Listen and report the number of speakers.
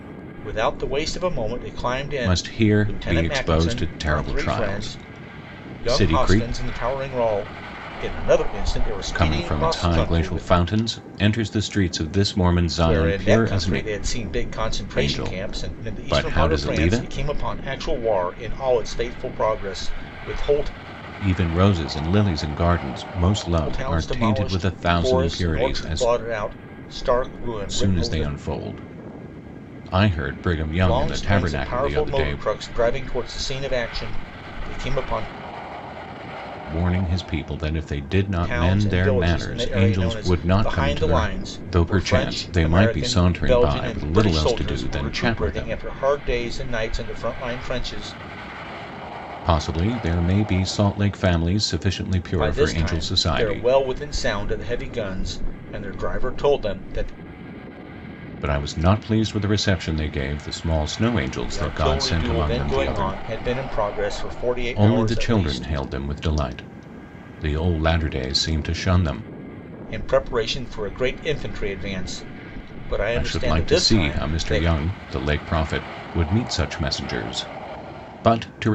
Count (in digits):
2